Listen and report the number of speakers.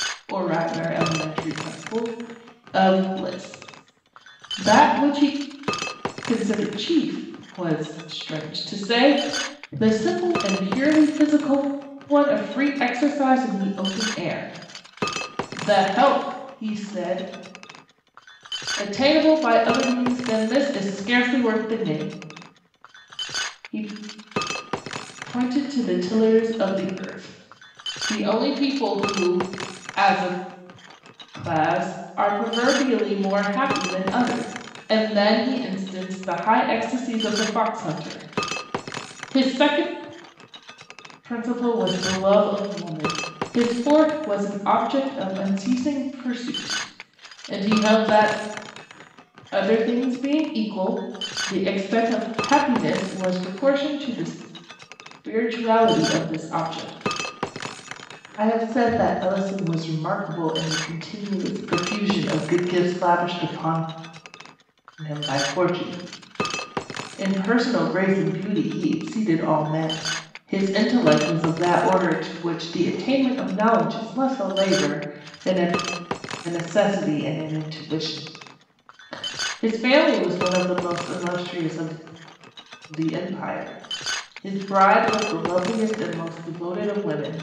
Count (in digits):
1